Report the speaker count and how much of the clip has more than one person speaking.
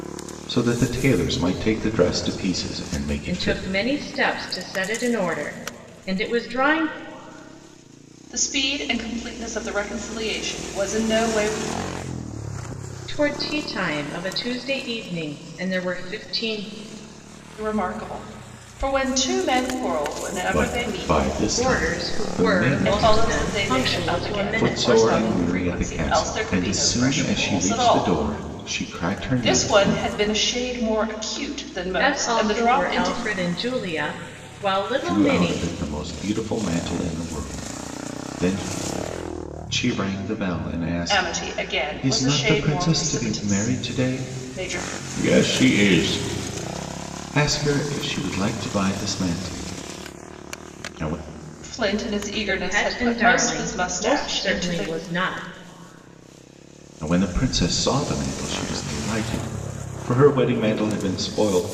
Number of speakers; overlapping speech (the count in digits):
3, about 27%